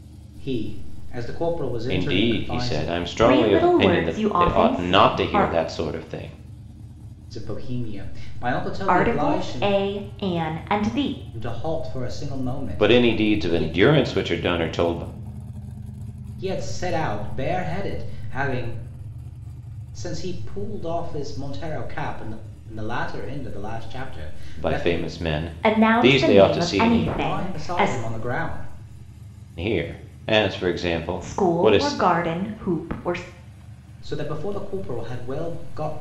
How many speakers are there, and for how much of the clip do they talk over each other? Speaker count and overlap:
three, about 24%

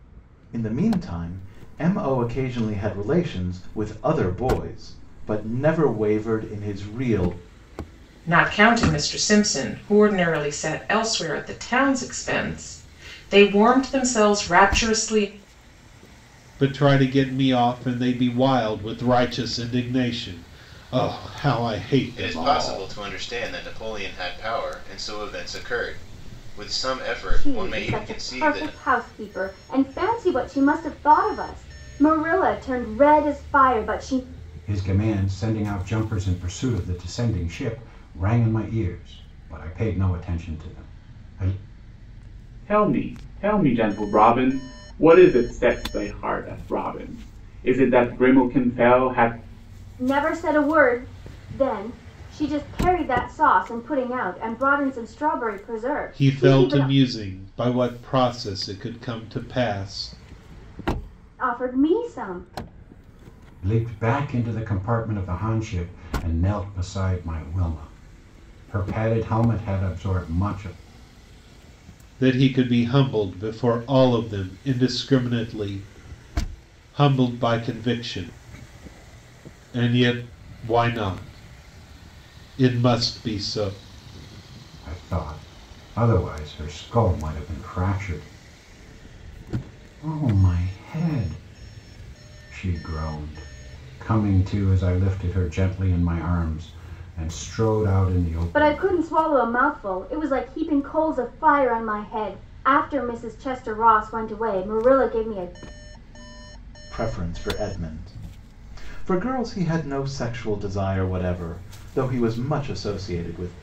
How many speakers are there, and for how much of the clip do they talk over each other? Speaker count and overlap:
seven, about 3%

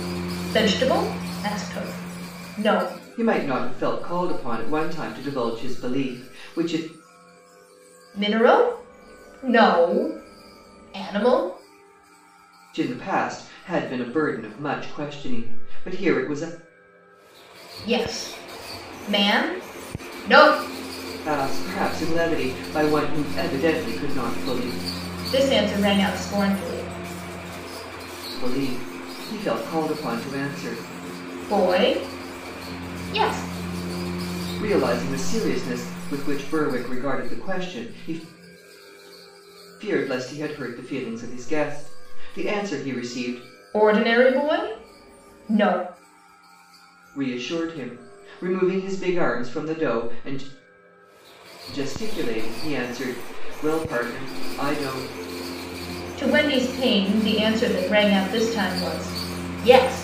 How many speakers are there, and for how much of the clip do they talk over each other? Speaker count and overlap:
two, no overlap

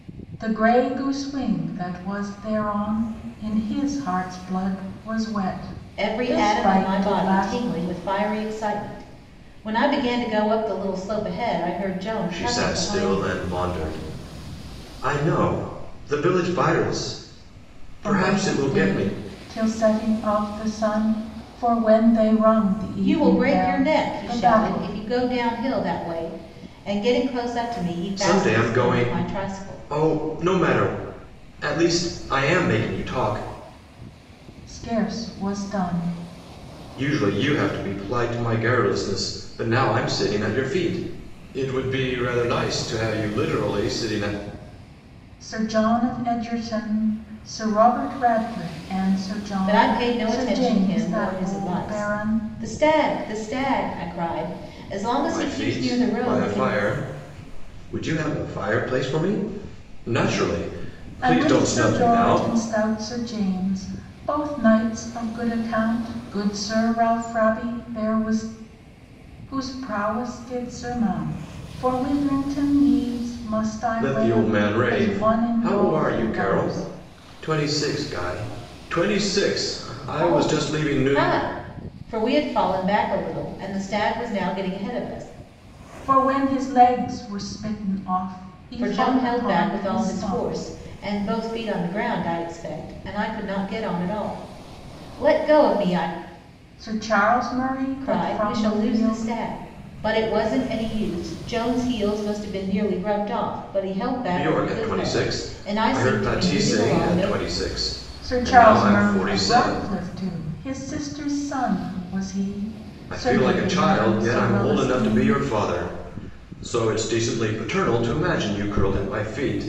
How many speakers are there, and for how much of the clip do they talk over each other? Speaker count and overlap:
three, about 23%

